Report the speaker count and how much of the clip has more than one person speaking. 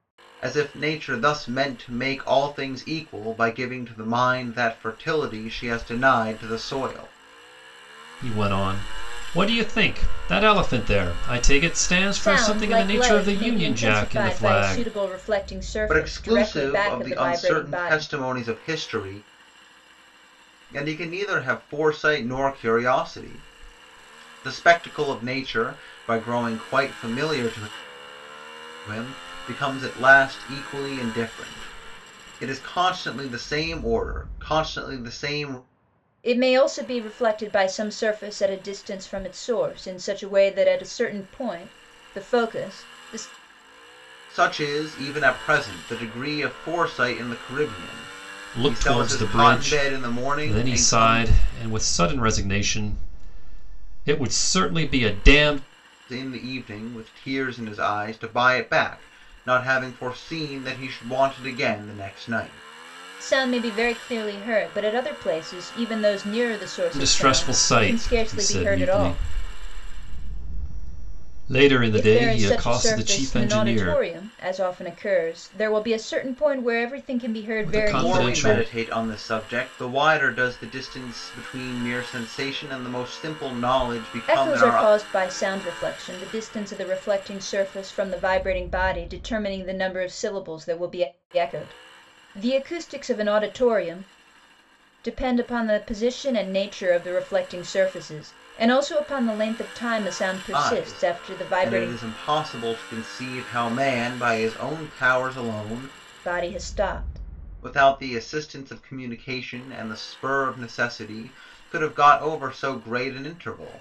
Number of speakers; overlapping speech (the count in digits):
3, about 14%